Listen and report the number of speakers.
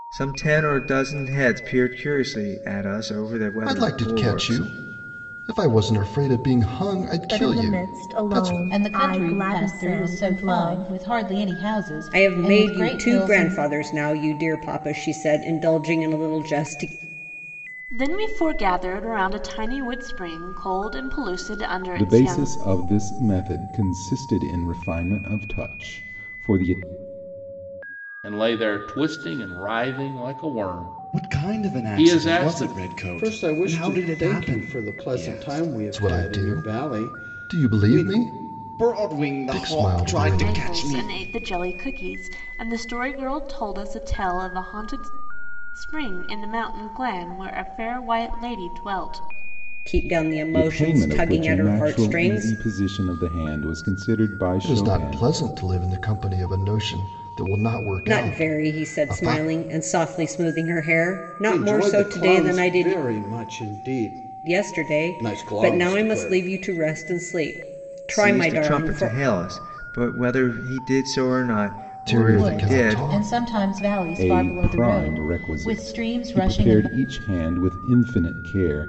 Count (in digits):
10